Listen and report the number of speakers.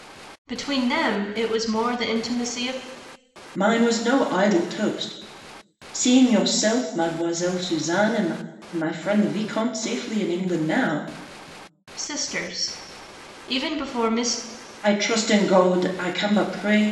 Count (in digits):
2